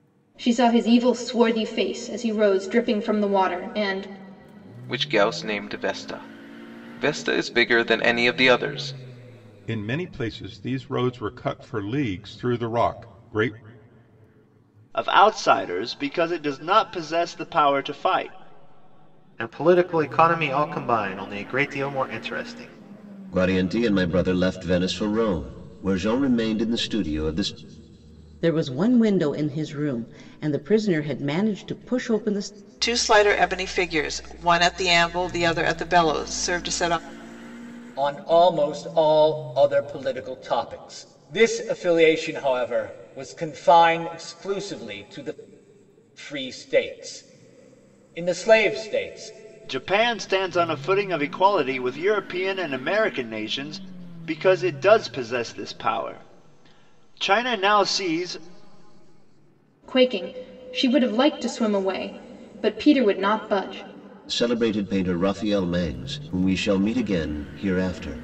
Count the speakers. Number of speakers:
9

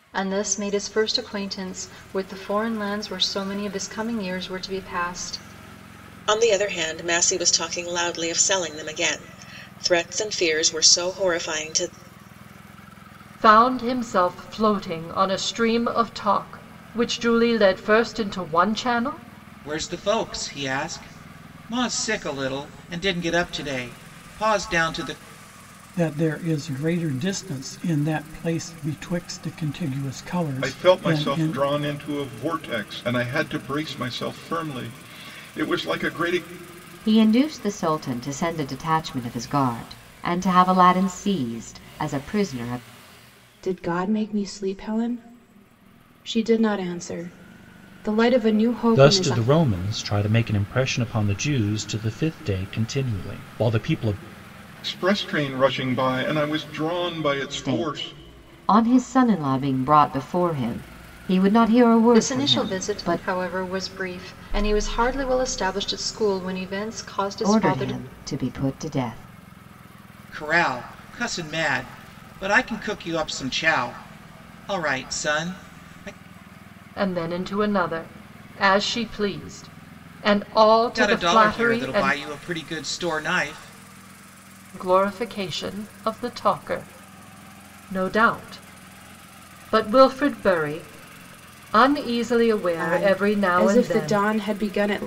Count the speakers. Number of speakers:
9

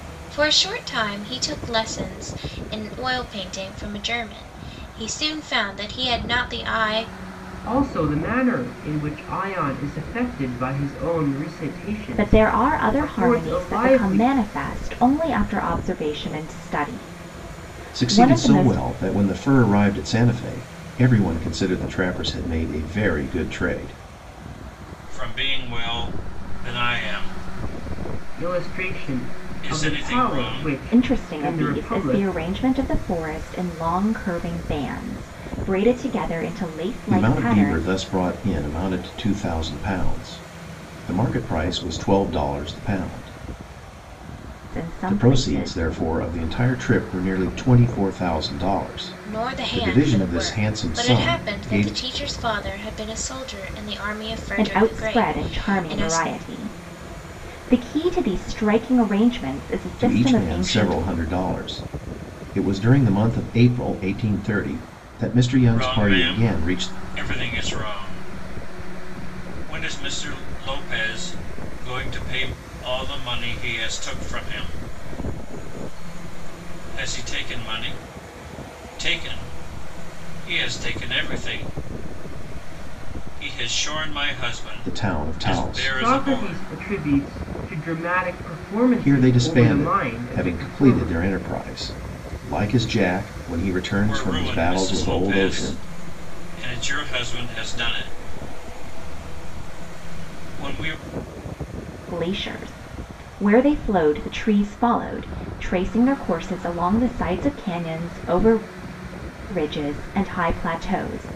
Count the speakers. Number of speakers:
5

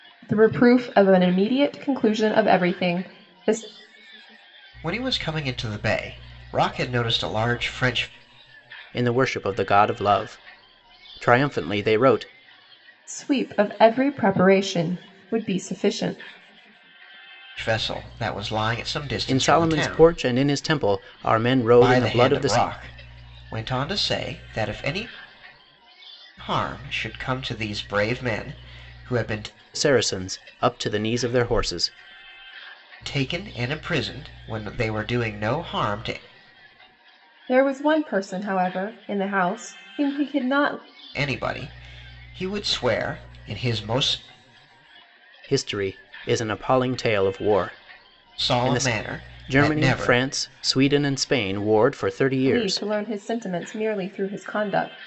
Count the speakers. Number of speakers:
3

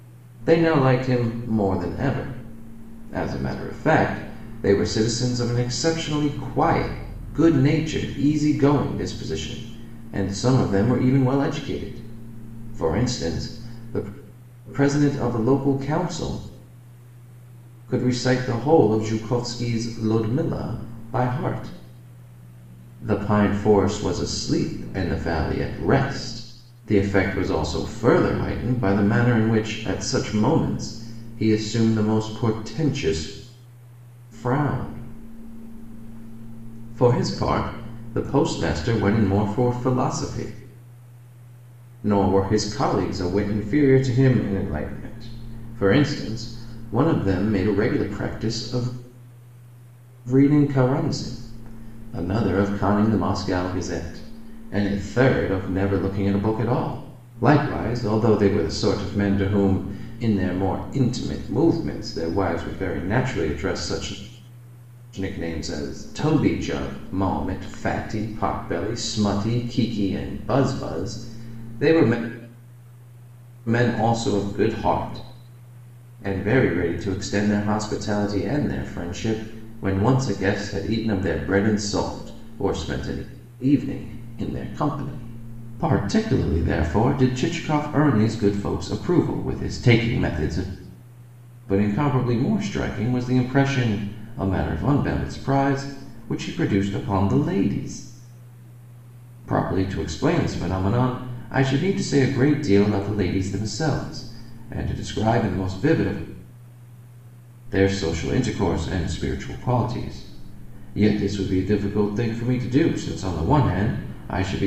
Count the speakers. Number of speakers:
1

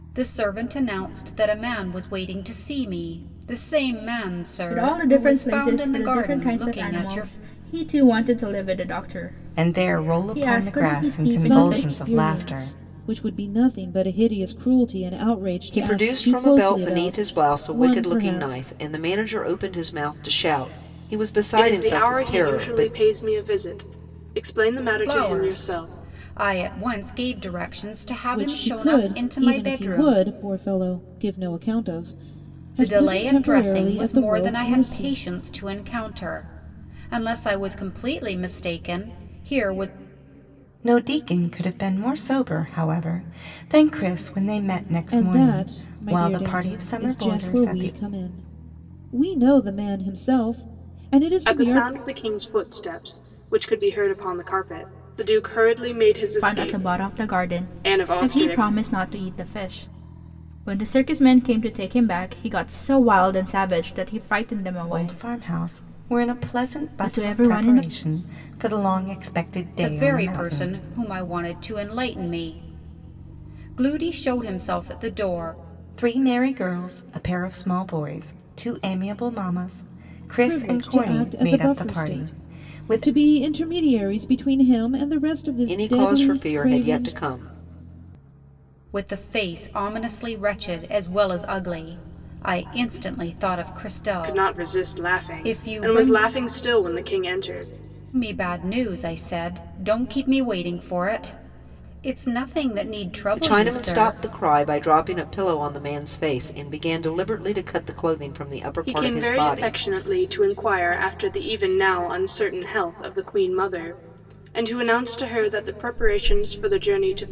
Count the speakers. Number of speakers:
6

